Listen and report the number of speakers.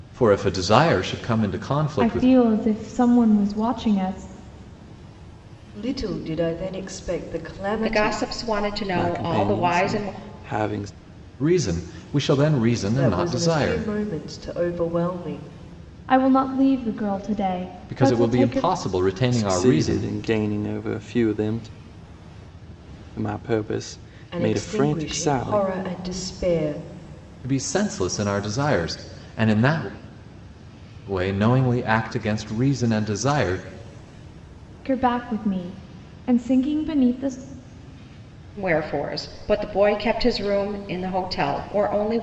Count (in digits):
5